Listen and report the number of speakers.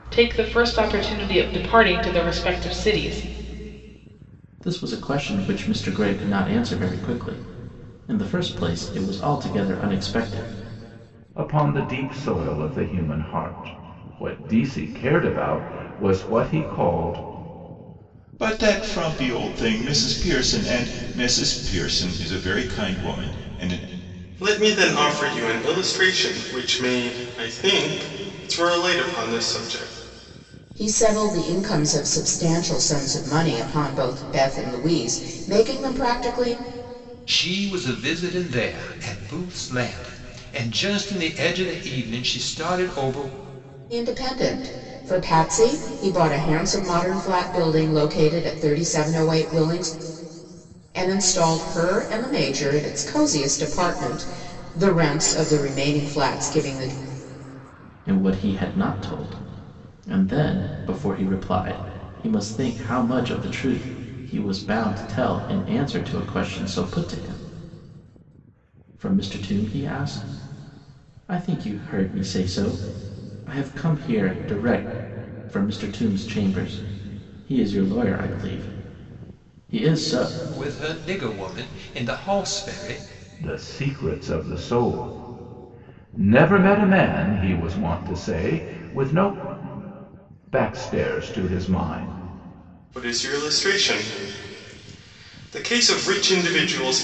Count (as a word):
seven